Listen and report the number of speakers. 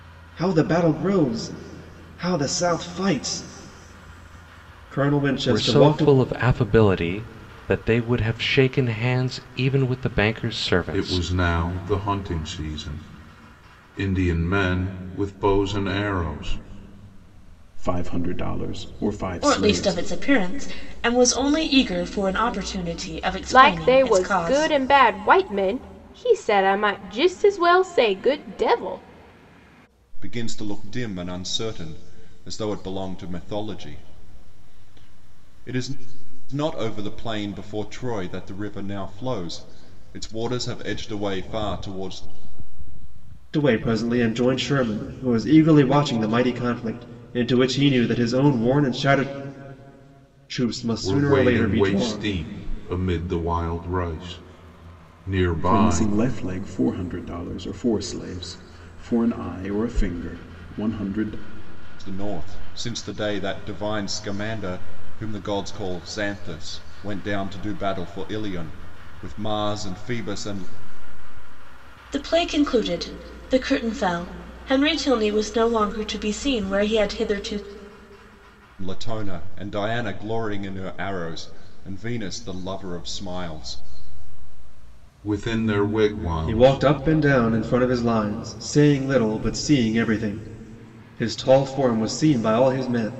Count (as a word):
seven